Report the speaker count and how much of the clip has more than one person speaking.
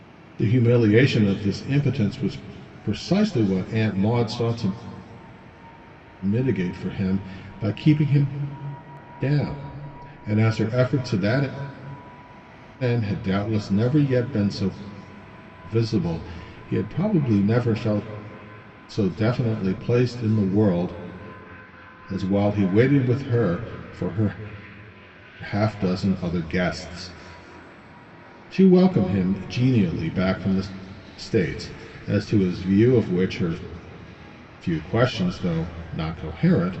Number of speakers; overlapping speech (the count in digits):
1, no overlap